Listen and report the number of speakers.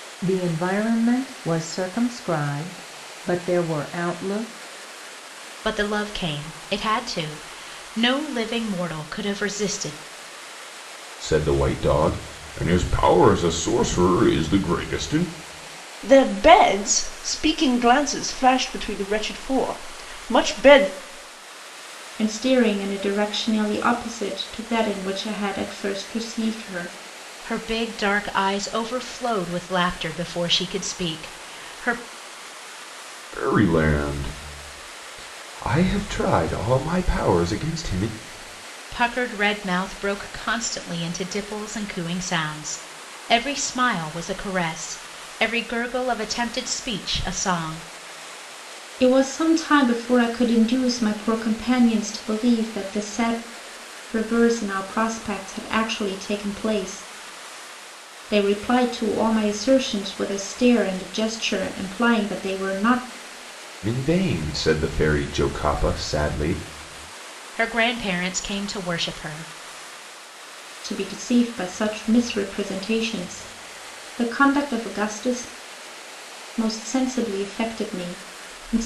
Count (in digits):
5